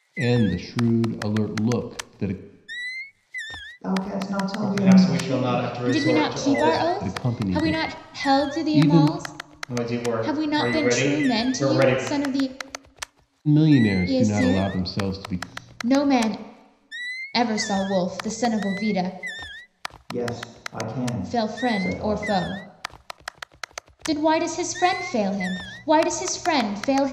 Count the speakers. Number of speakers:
4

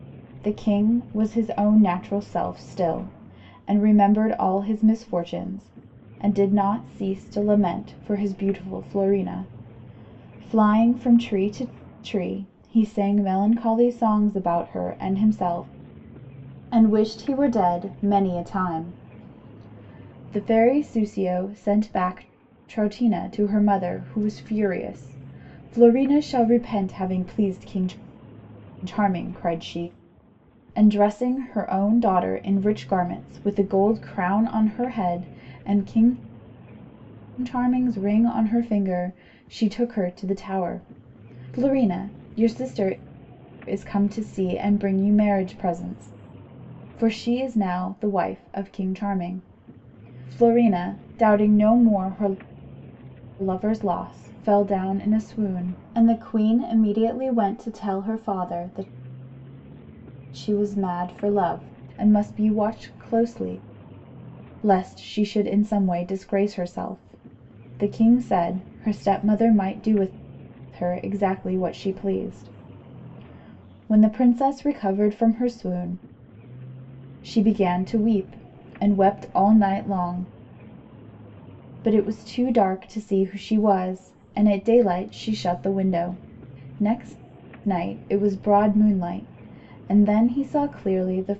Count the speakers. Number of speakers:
1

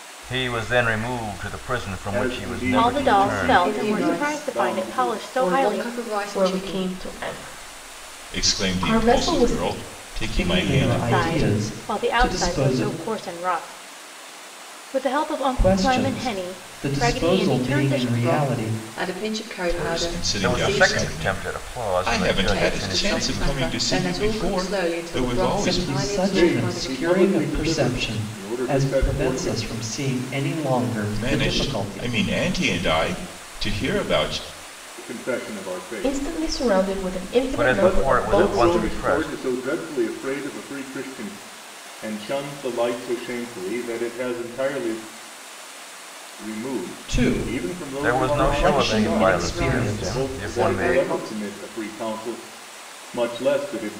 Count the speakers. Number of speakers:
7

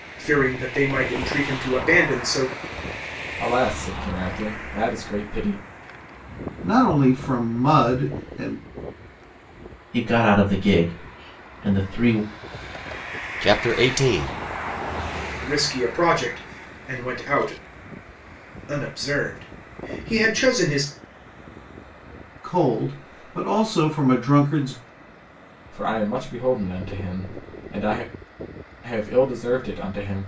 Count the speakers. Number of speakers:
5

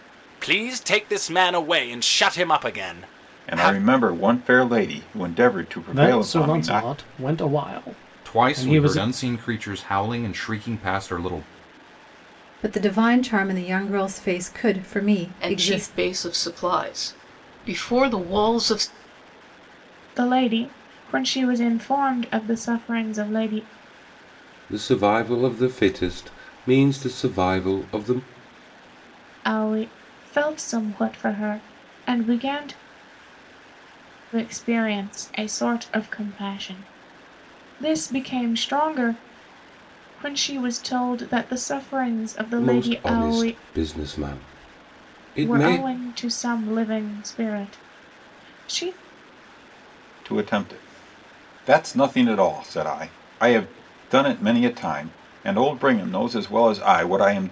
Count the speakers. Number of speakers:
8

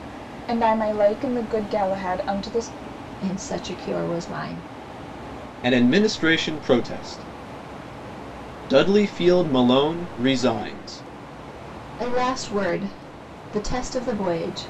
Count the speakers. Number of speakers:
3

